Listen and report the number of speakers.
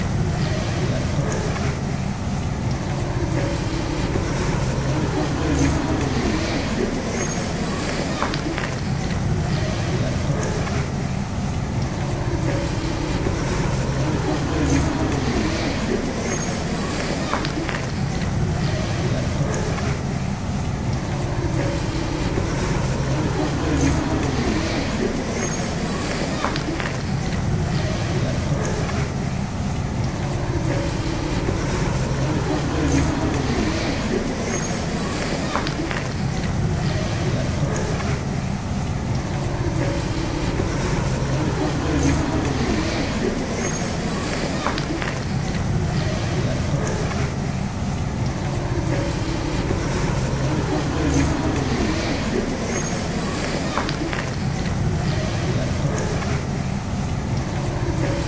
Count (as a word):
zero